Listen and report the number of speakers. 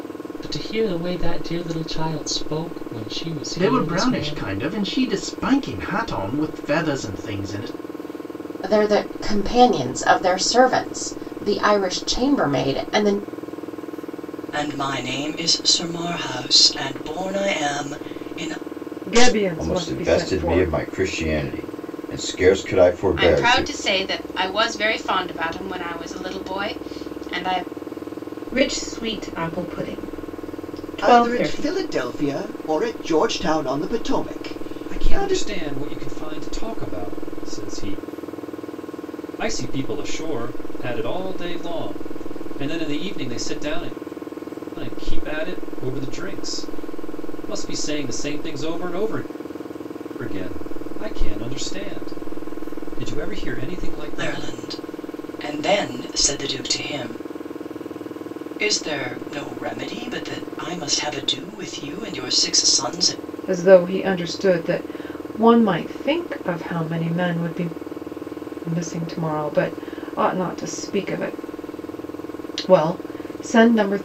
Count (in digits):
10